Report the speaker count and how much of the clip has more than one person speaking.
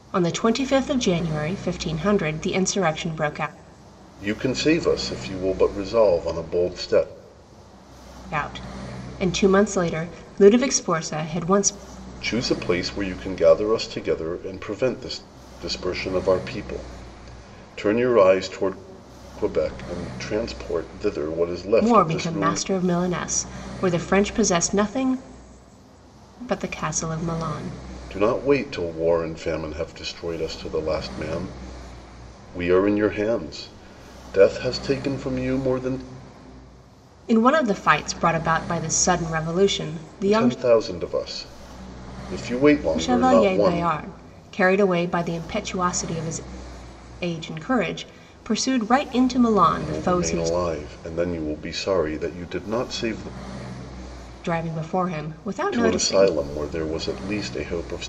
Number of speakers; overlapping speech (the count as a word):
two, about 6%